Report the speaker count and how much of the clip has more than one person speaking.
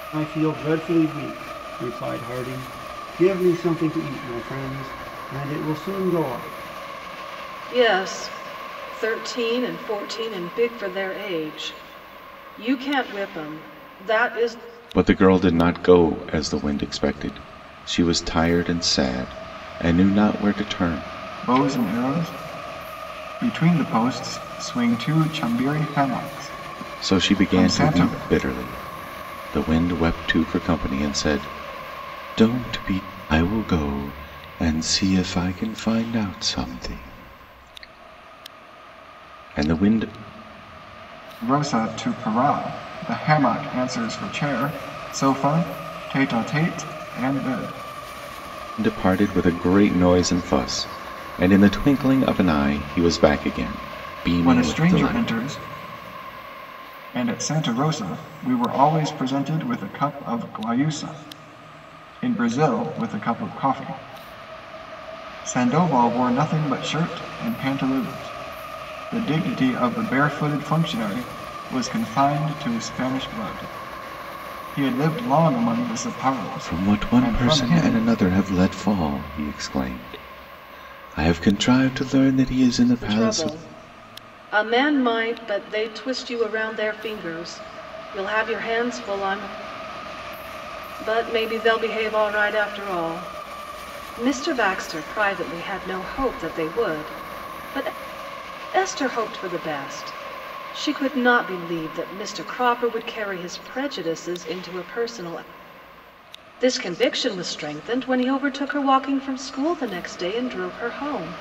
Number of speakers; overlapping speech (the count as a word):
four, about 4%